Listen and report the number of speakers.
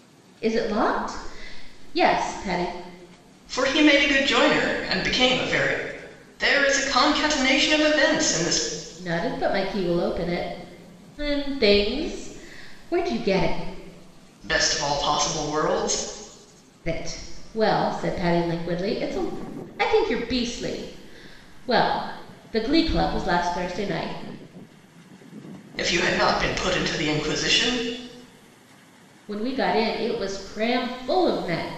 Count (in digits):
2